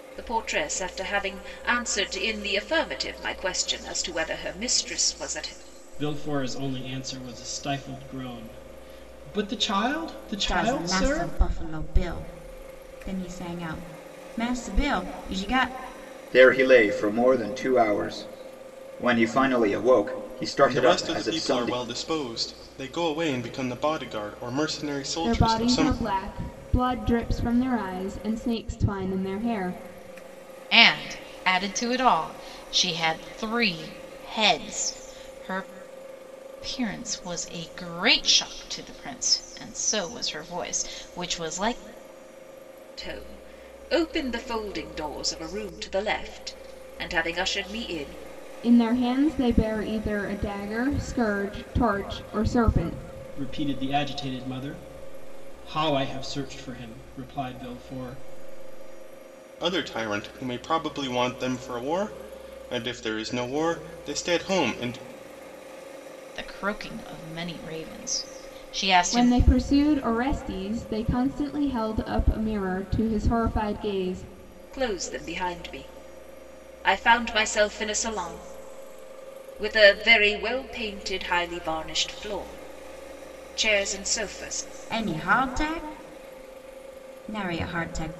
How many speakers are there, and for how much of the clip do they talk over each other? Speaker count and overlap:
7, about 4%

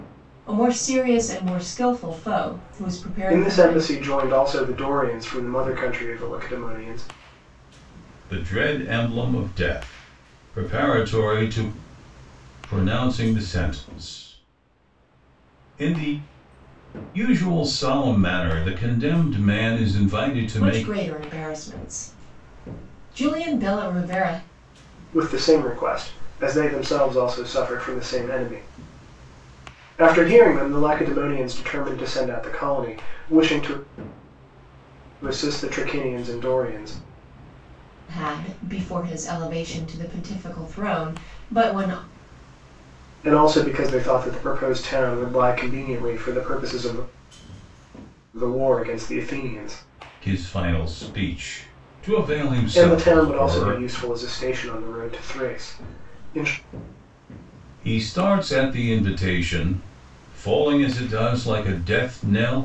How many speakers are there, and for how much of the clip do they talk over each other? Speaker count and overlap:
3, about 3%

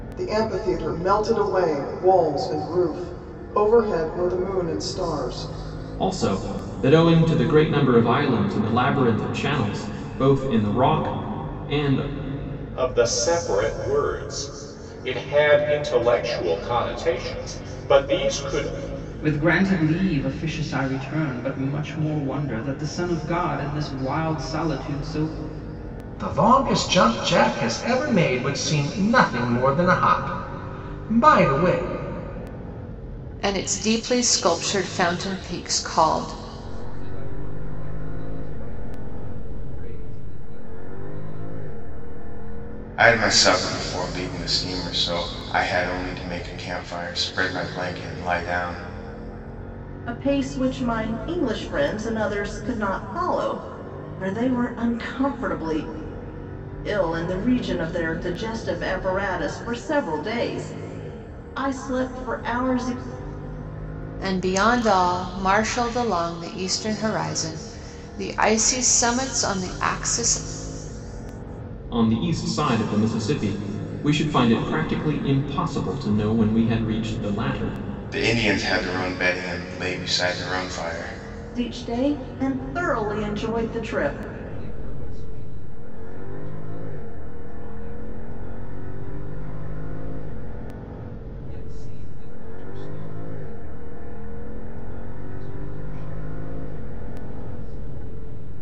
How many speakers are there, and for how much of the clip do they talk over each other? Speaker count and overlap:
9, no overlap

